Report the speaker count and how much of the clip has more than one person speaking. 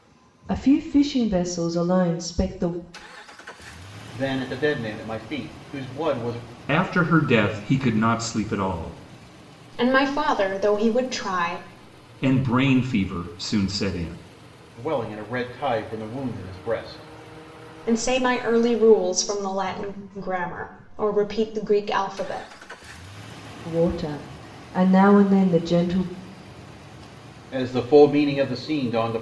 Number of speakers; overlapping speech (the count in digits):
4, no overlap